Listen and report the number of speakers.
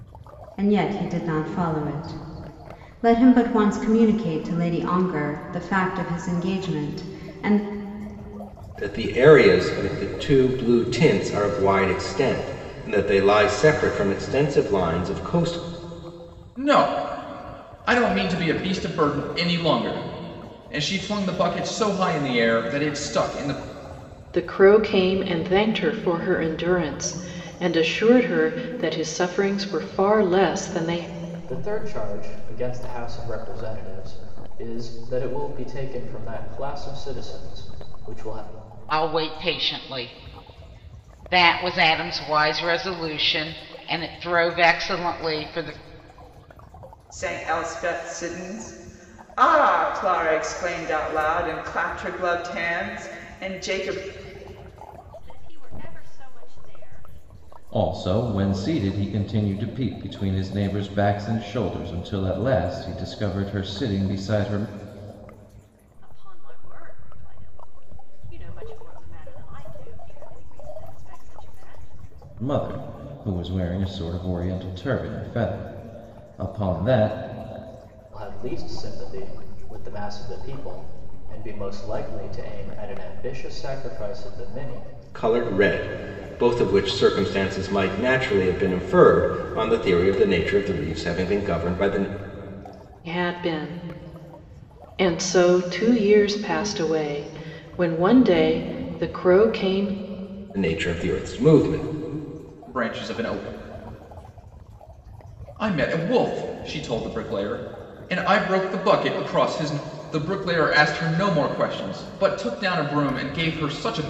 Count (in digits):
9